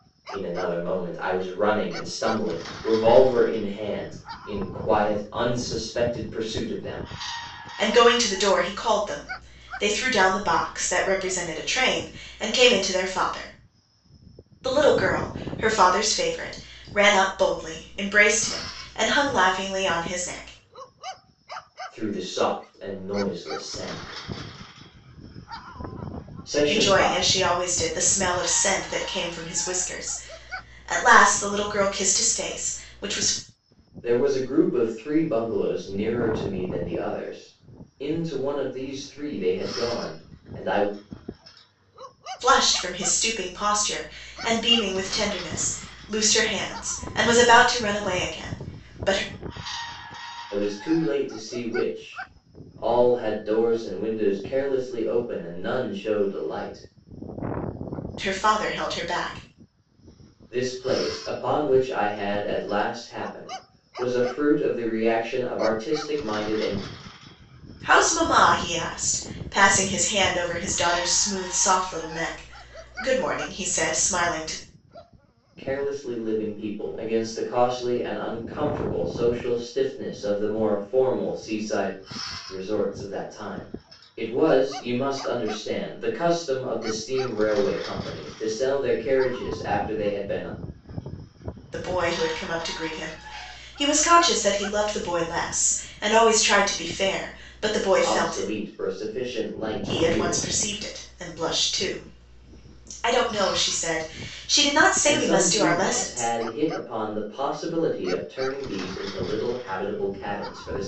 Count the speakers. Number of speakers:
two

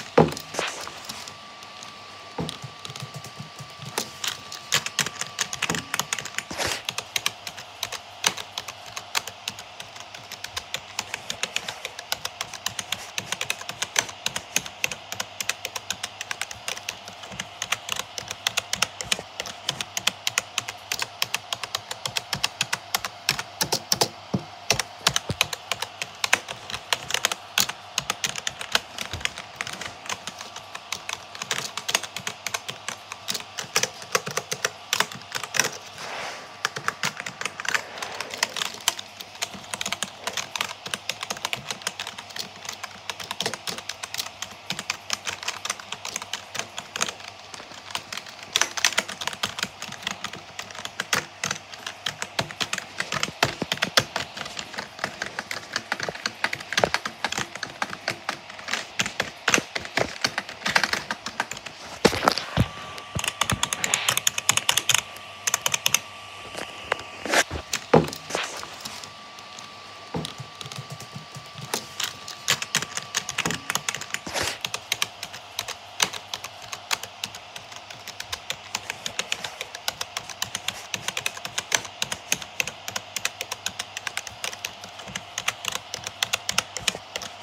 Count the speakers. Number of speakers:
zero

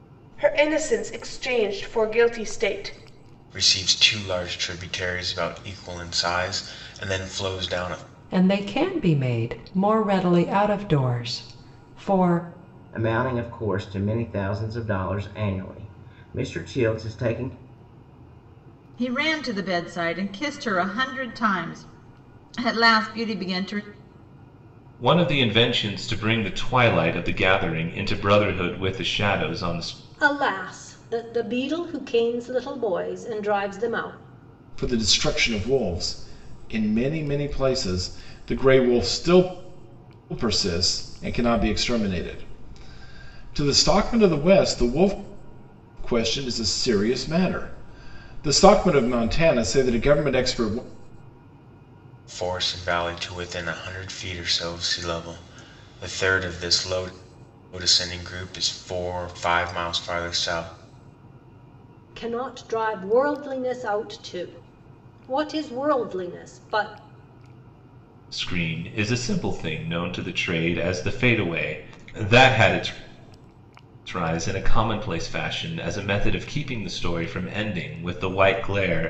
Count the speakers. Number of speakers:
eight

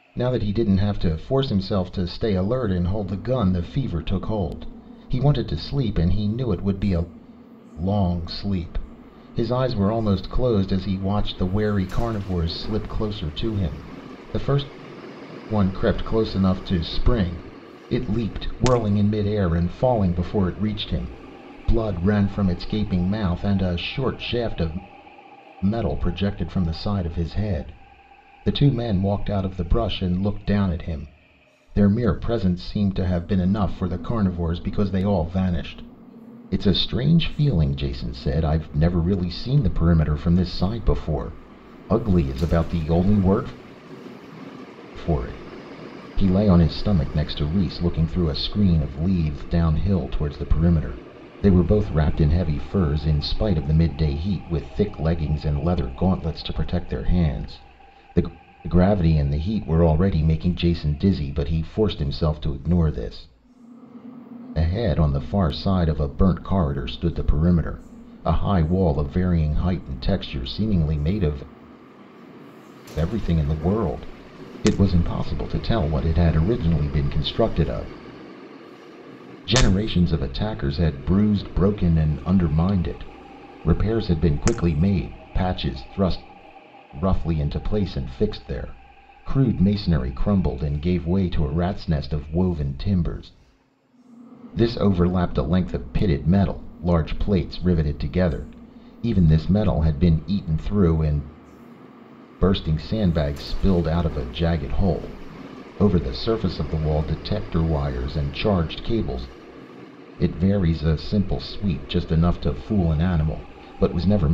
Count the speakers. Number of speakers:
one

